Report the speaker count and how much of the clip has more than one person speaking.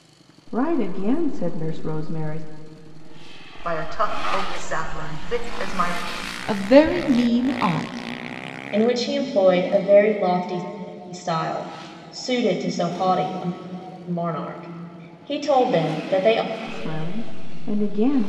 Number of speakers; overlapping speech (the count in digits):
4, no overlap